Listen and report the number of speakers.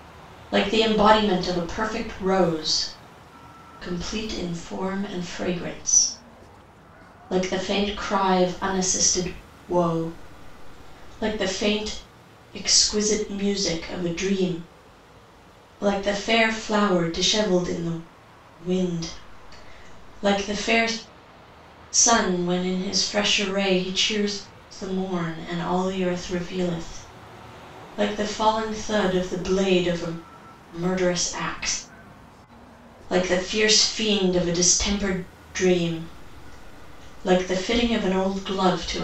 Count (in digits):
1